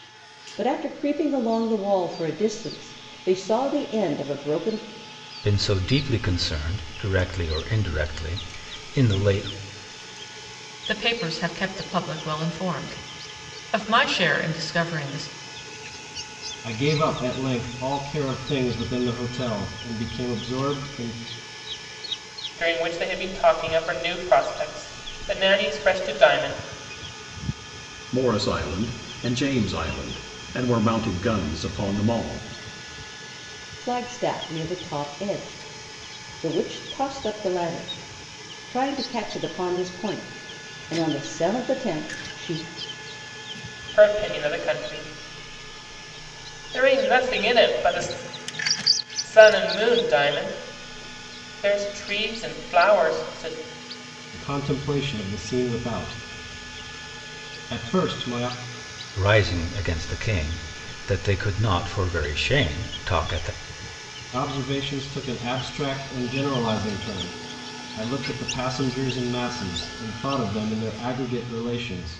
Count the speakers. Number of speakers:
six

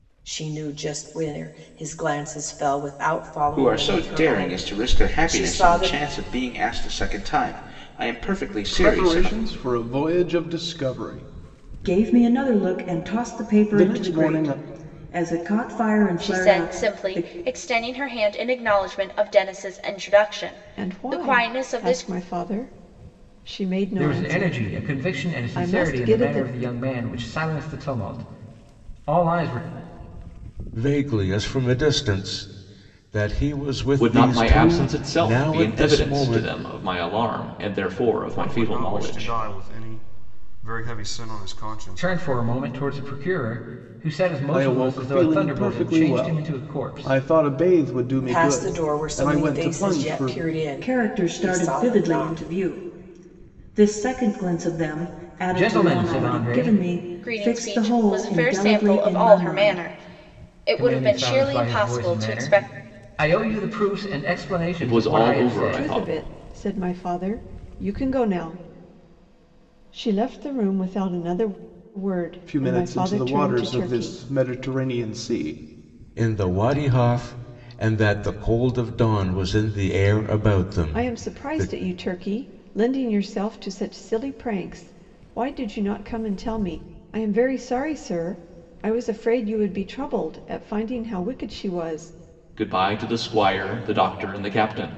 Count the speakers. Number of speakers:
ten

